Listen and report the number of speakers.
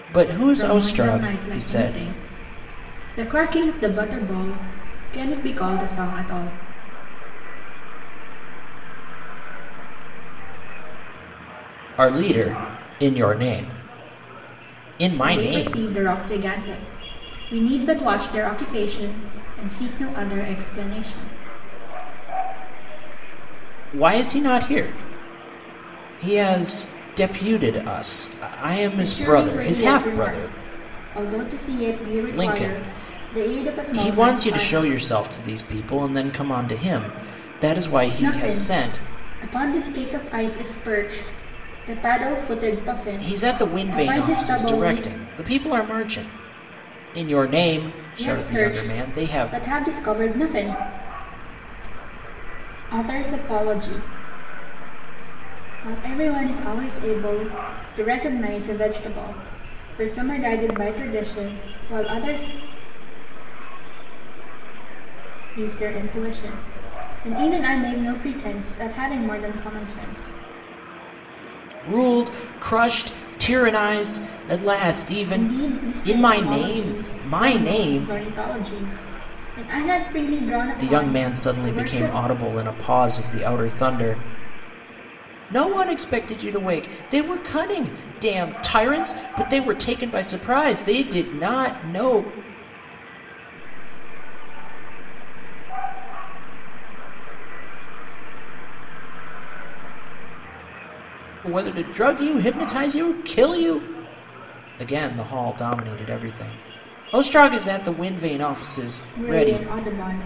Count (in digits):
3